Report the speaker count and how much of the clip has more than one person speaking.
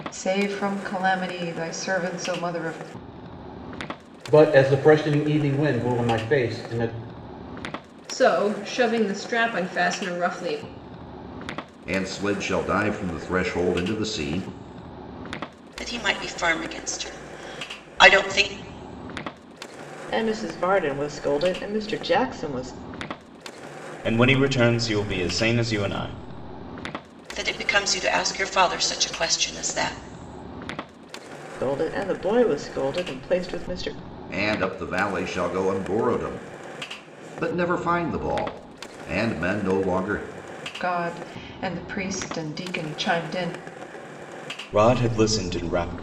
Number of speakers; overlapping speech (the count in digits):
7, no overlap